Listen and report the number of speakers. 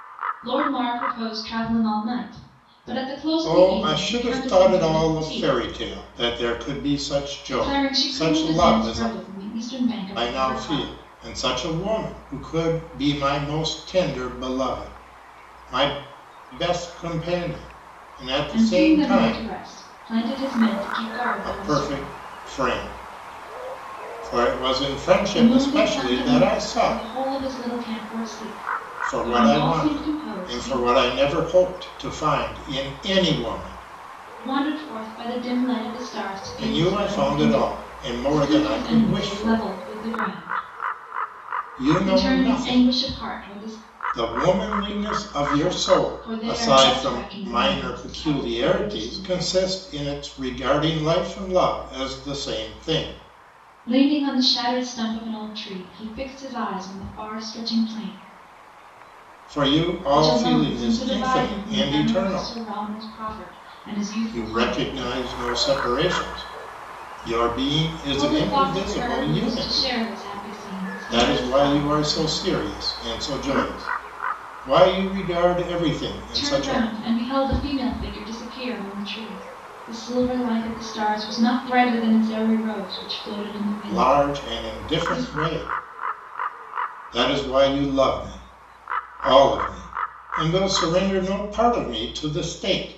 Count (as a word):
two